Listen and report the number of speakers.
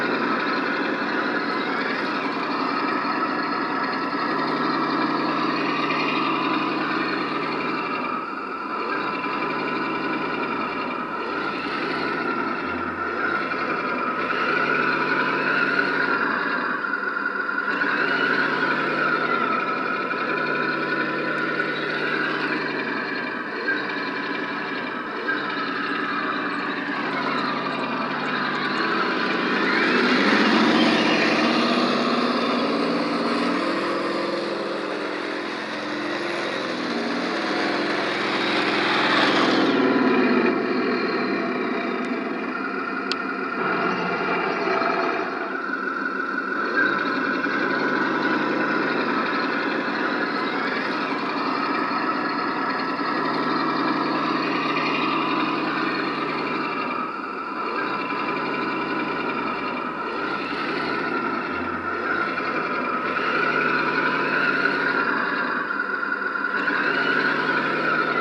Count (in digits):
0